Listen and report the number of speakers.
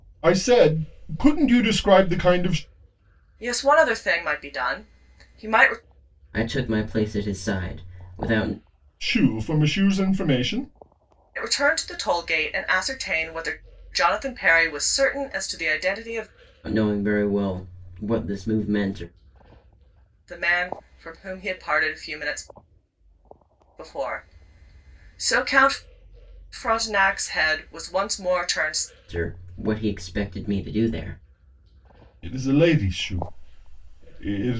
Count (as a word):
three